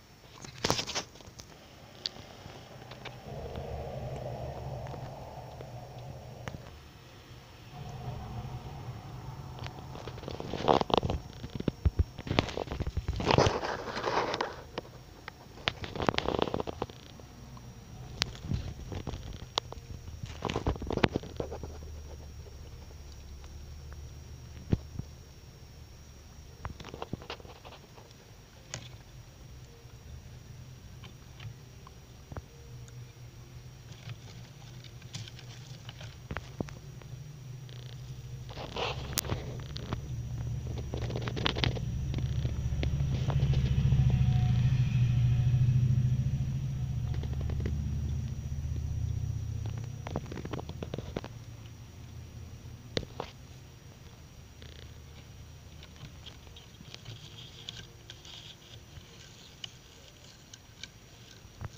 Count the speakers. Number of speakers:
0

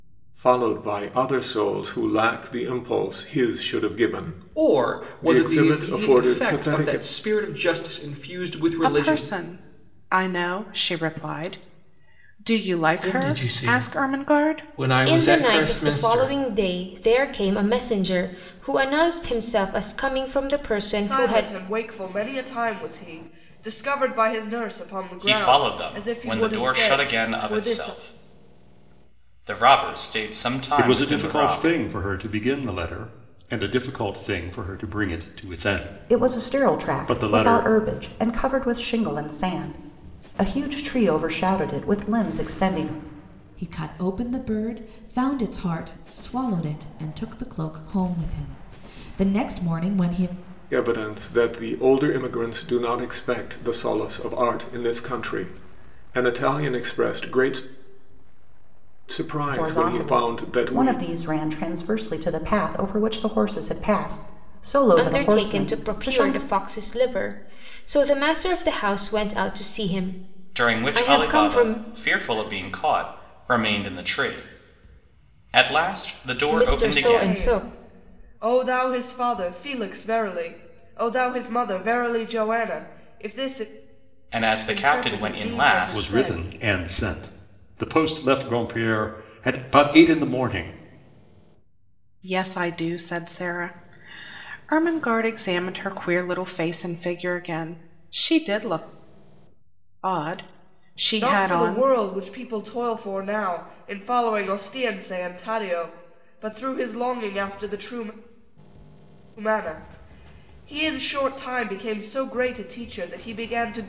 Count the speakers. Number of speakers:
10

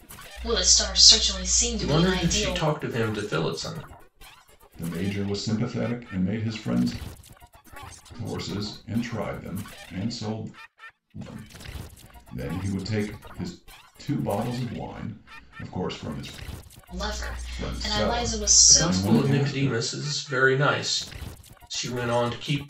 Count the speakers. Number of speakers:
3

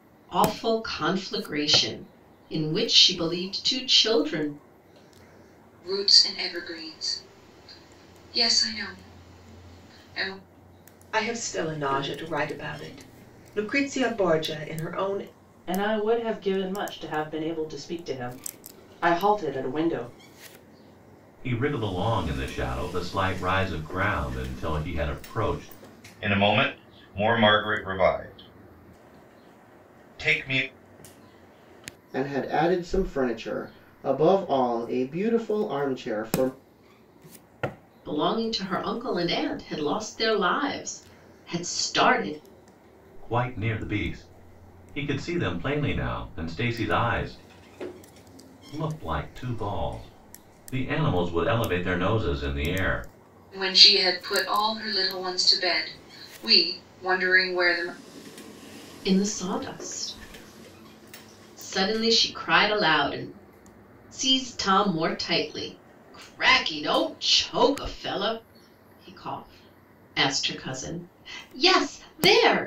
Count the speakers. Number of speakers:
7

